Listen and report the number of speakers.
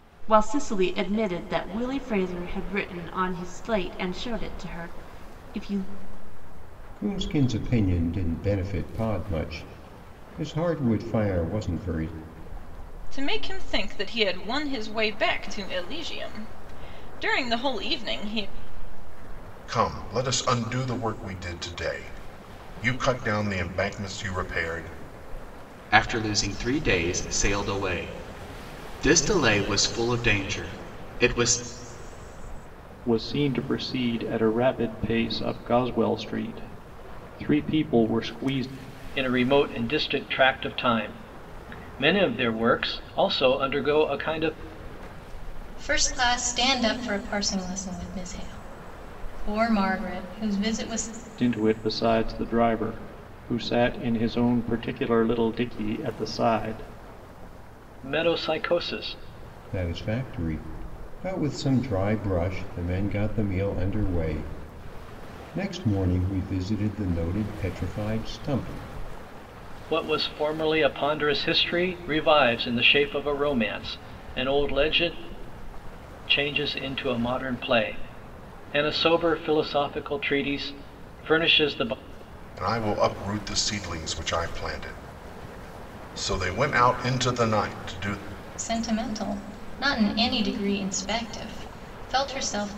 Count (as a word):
eight